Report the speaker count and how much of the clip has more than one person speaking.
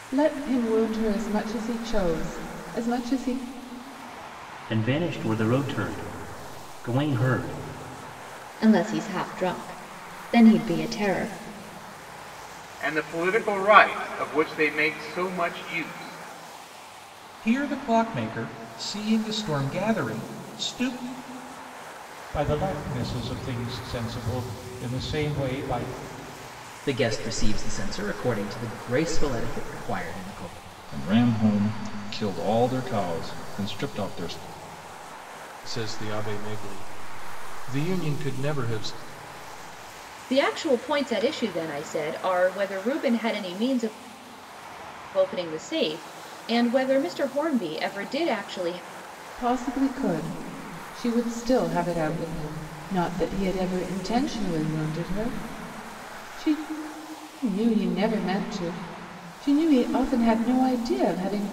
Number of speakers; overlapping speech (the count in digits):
10, no overlap